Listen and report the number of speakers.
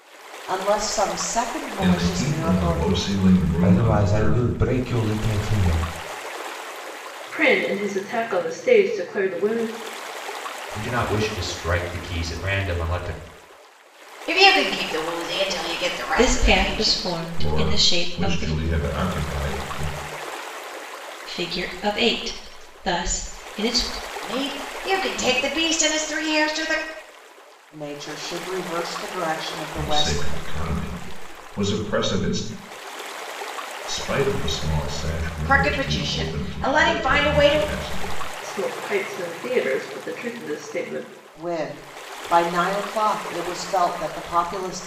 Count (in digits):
7